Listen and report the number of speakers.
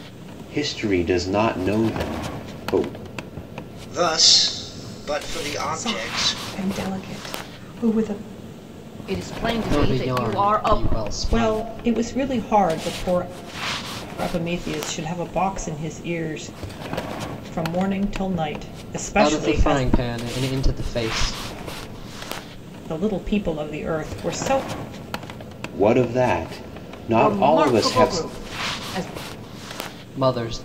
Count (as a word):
six